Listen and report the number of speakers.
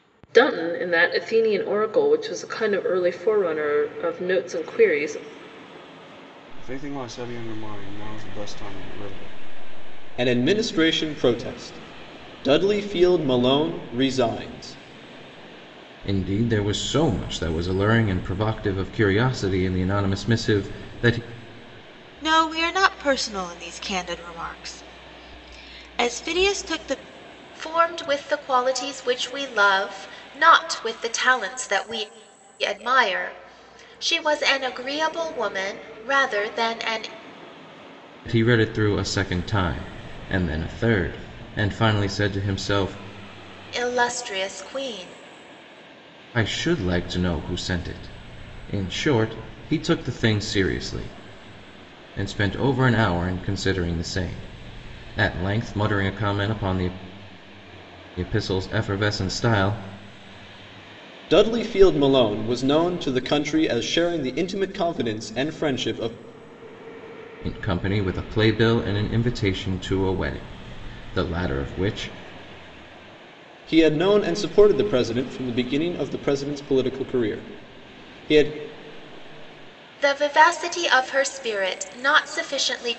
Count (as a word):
six